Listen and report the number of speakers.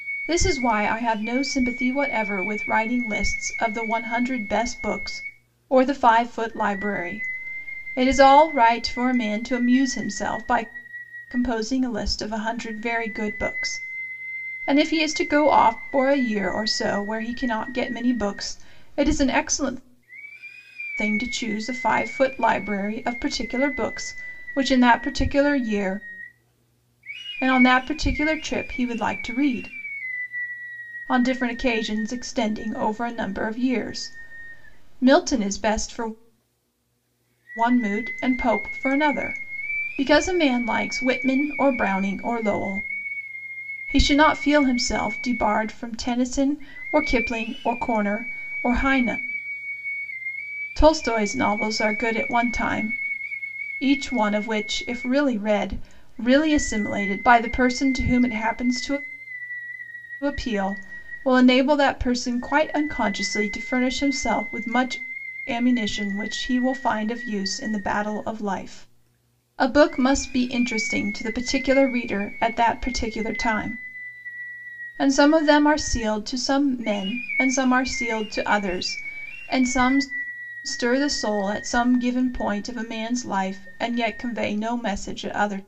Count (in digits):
1